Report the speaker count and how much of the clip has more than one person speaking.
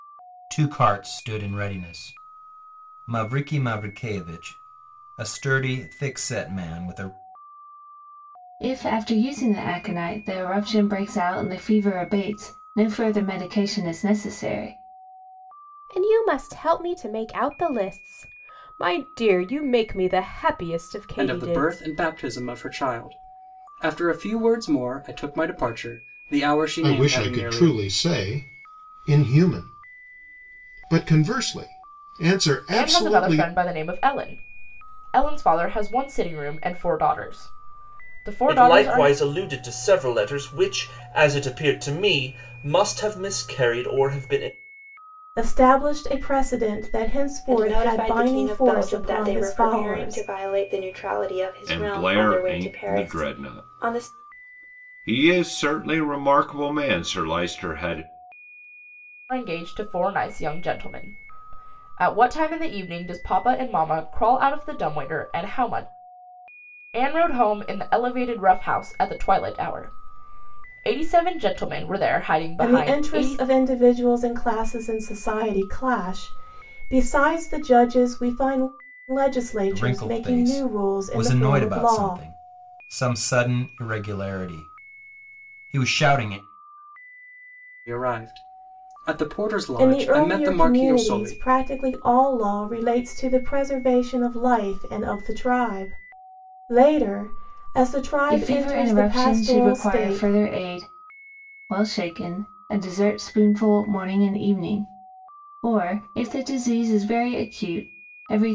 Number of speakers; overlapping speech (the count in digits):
10, about 14%